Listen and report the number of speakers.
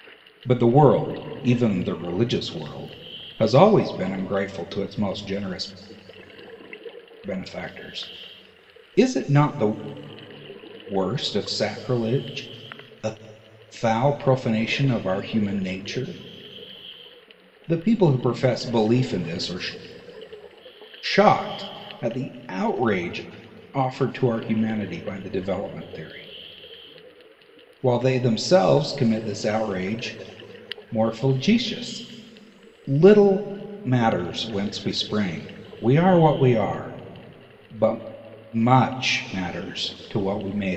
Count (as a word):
one